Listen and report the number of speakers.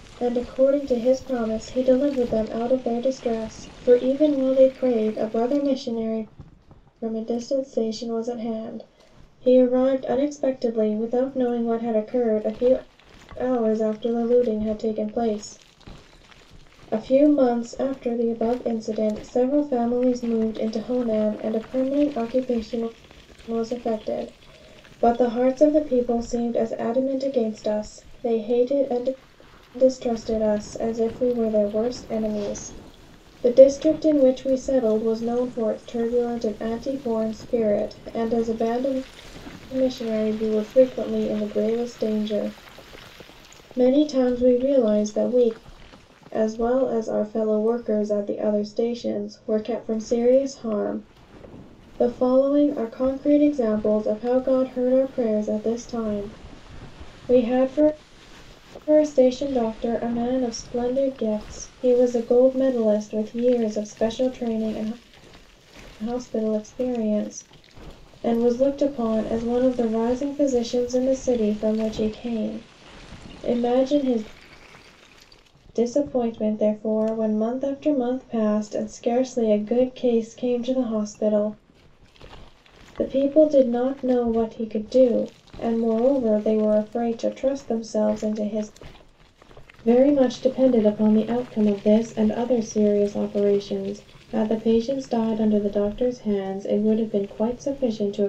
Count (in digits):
1